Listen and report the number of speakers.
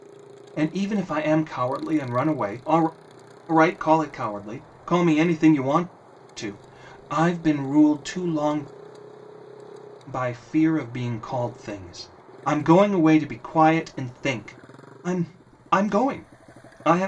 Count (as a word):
one